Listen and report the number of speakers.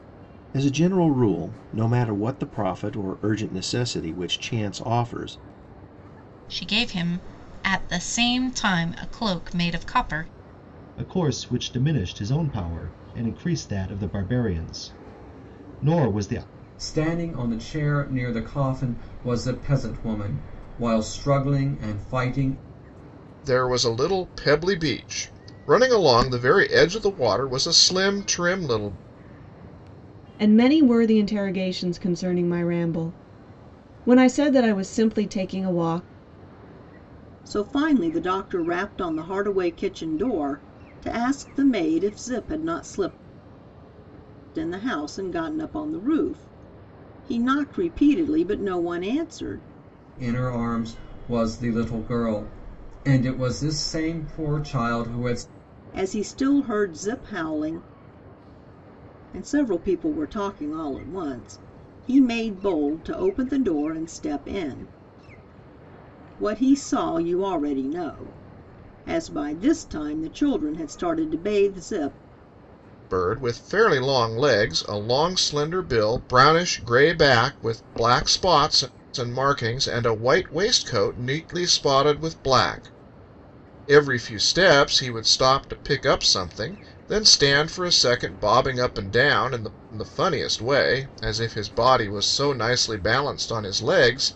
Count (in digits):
7